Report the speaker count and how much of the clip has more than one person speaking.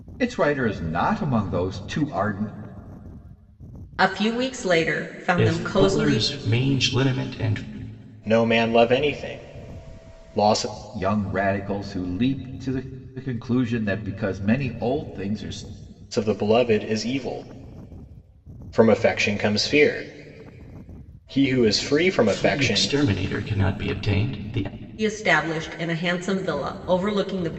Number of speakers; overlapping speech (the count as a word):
four, about 5%